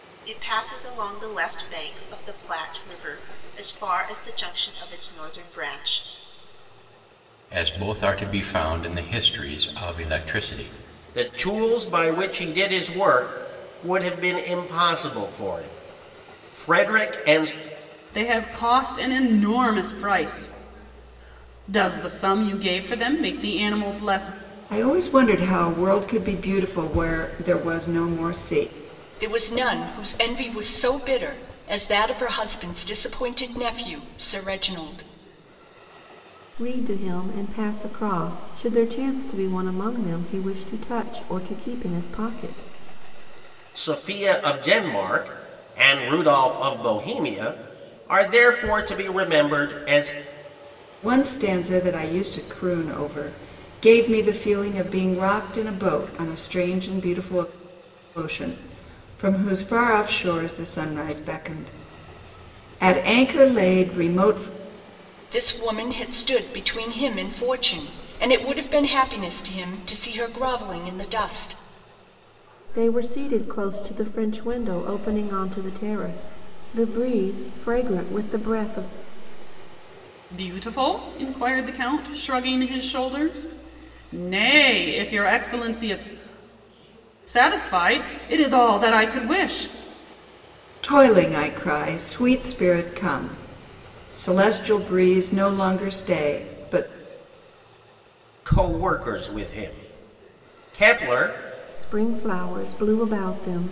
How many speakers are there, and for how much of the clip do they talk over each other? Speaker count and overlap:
7, no overlap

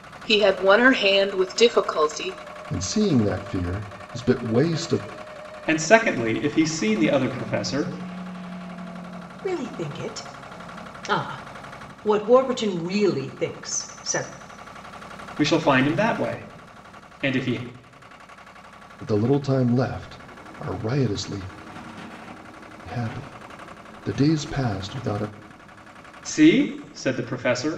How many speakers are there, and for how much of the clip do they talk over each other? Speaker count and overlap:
4, no overlap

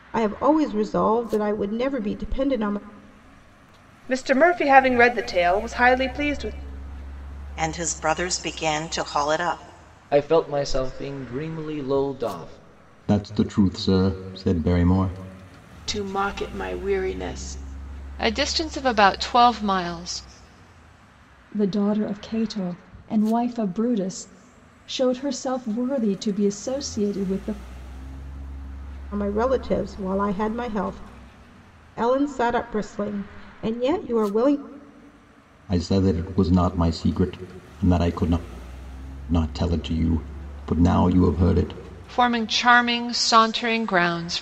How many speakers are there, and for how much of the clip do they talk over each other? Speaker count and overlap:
8, no overlap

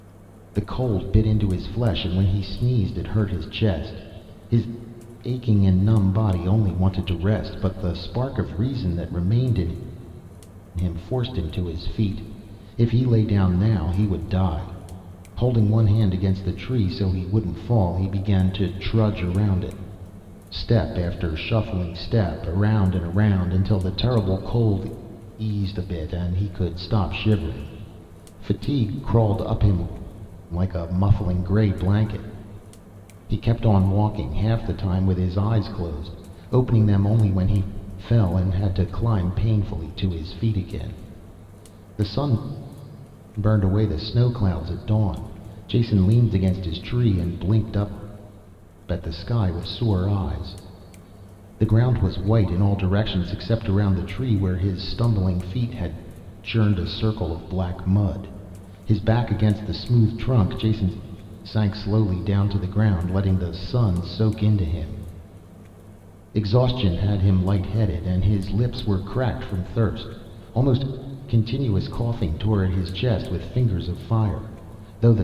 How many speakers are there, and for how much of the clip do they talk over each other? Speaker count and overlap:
1, no overlap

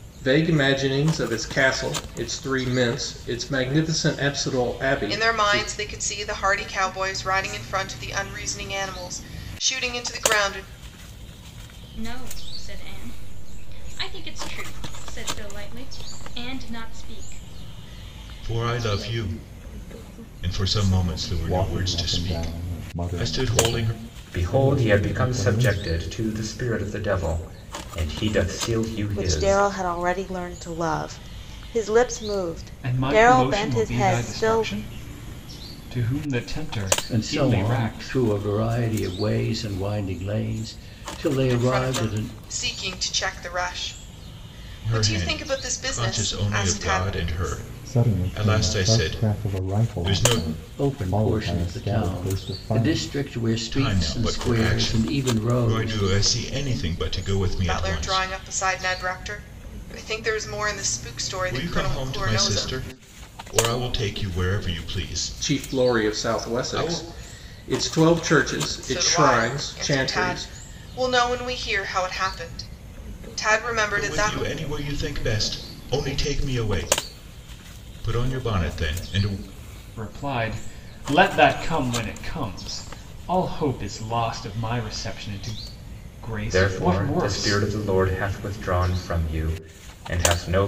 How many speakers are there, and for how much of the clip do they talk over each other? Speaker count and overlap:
9, about 29%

